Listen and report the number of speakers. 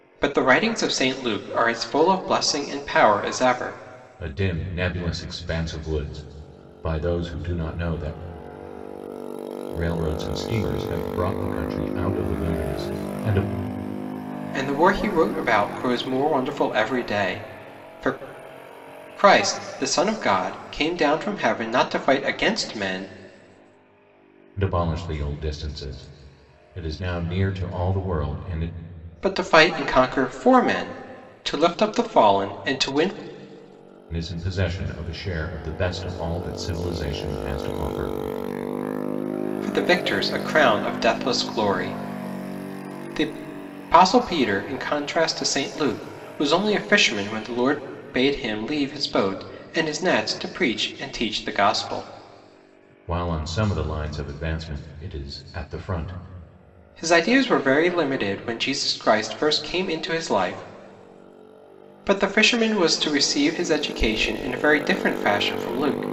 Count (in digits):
2